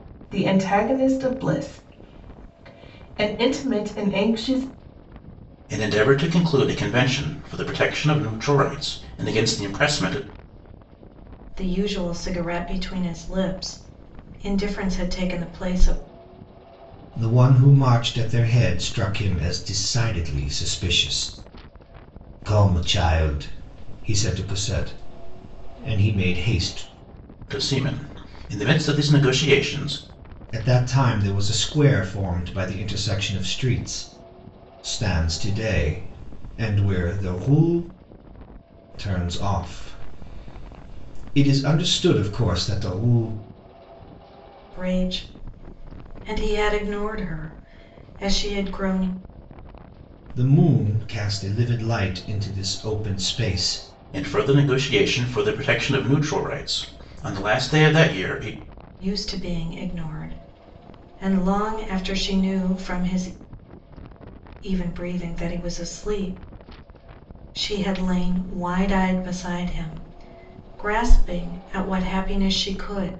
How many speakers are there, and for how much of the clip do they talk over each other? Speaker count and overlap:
4, no overlap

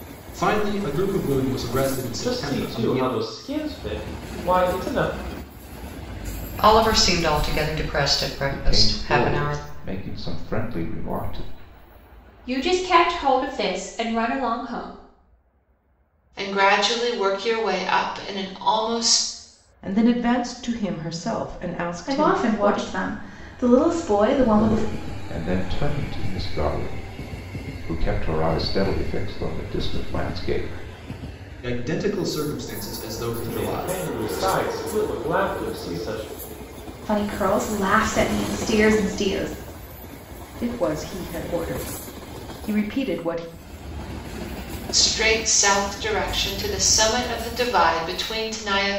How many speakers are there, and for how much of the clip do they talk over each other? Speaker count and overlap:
8, about 9%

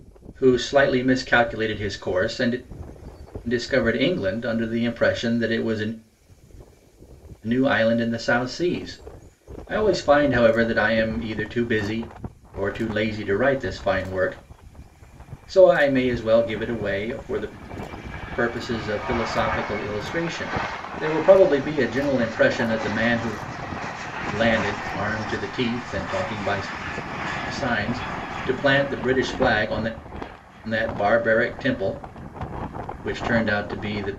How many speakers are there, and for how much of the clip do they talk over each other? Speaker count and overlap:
1, no overlap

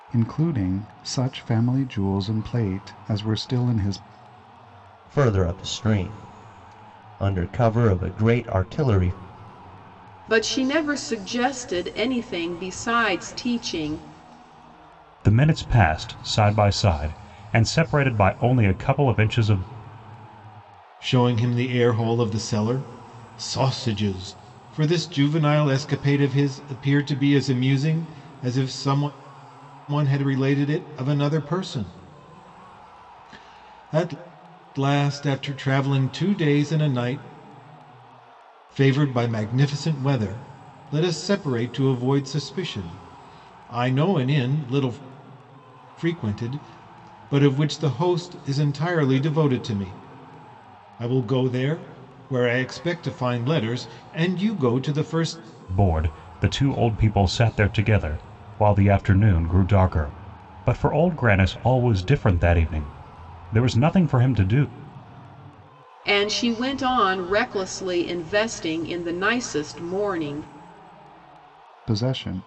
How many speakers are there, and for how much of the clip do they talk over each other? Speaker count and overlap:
5, no overlap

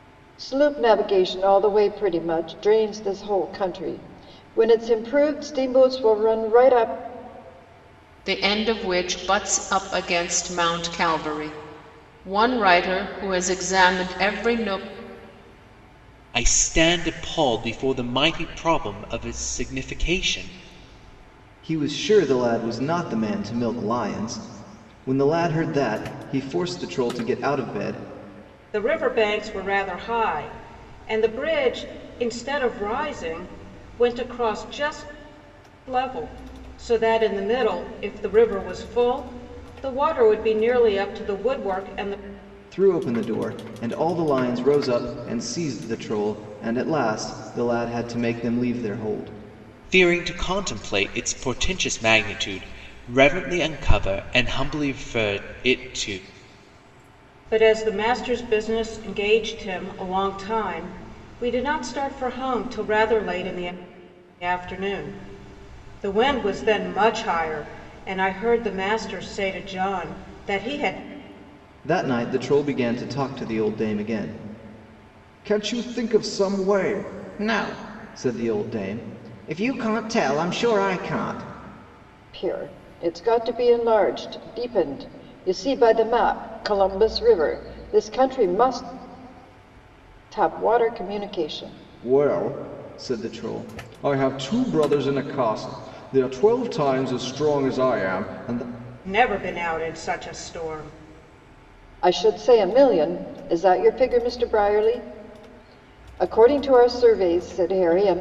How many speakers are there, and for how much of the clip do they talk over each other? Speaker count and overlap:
5, no overlap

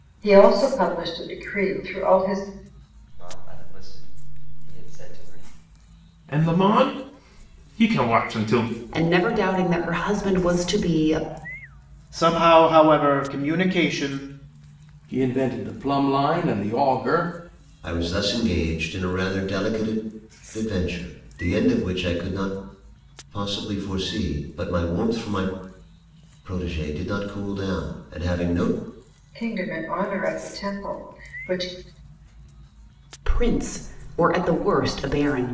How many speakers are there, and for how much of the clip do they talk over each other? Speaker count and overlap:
7, no overlap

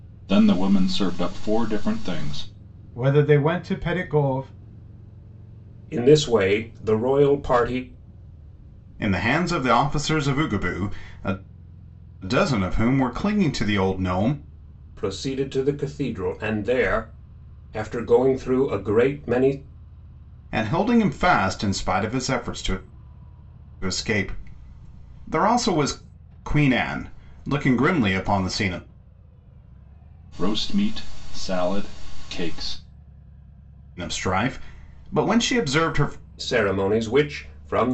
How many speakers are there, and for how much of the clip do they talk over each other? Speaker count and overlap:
3, no overlap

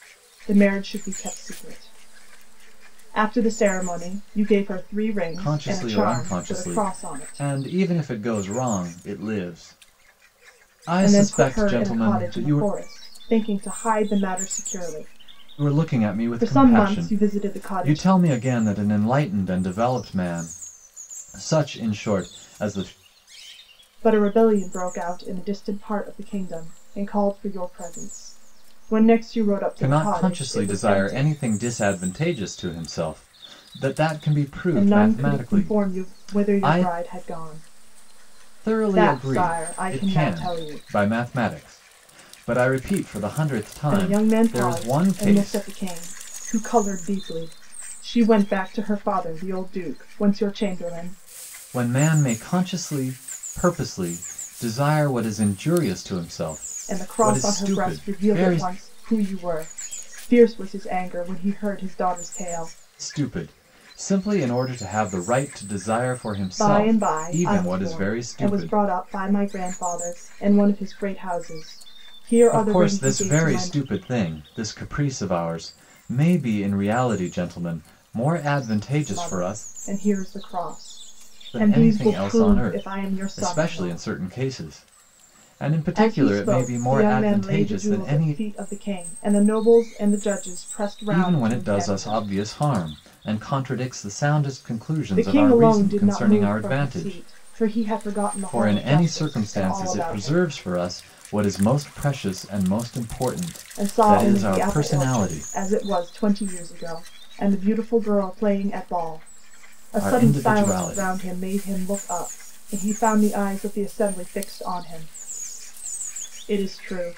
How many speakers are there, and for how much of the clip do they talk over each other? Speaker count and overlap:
2, about 29%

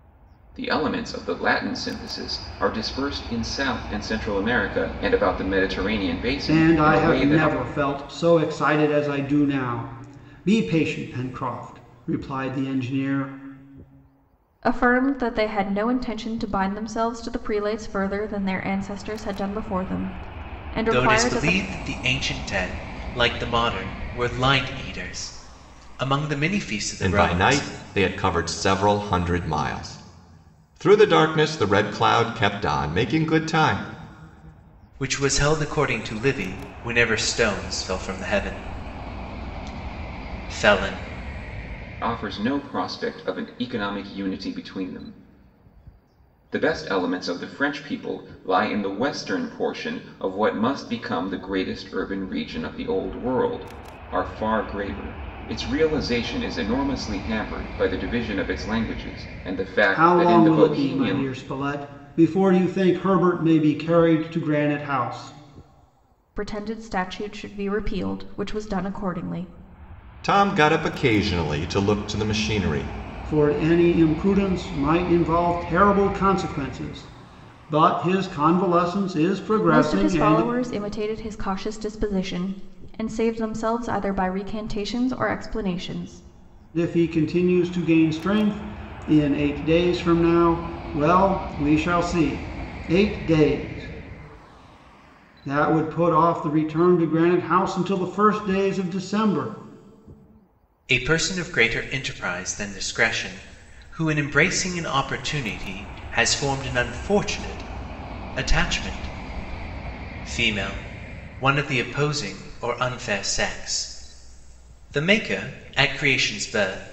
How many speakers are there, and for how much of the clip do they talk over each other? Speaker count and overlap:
5, about 4%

